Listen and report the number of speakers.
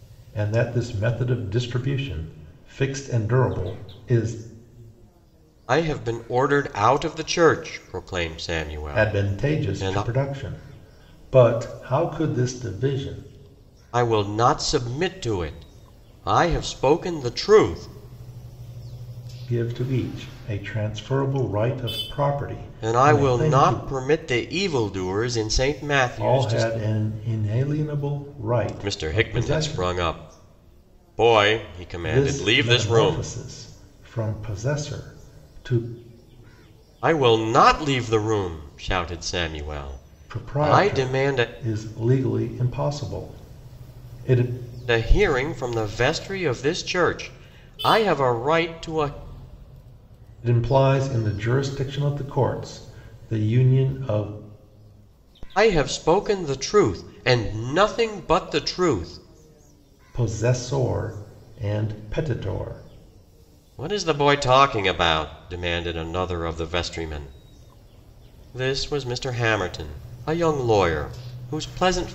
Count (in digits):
2